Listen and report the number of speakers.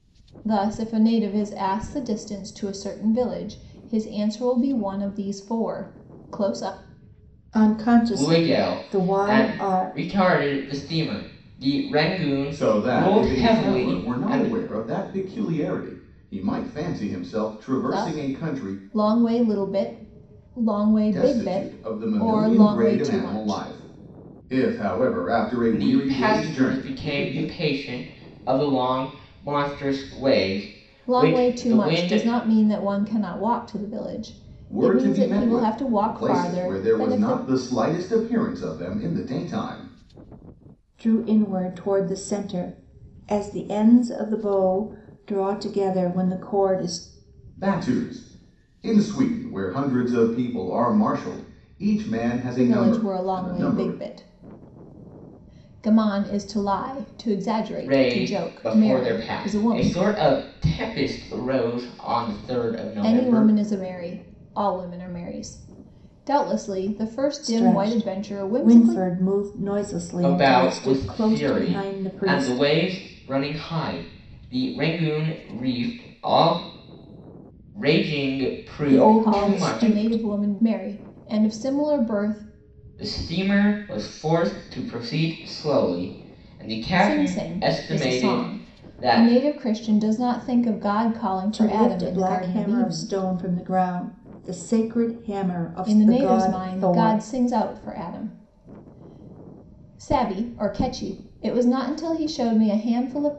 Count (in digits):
4